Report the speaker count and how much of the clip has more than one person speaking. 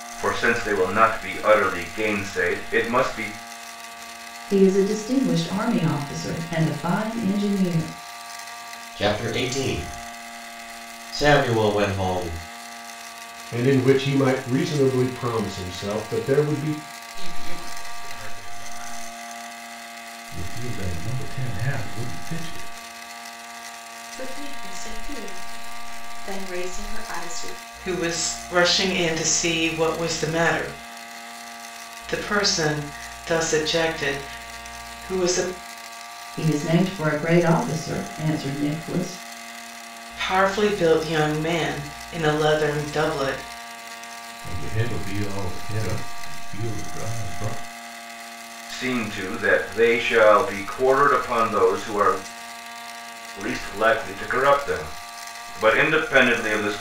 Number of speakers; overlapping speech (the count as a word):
eight, no overlap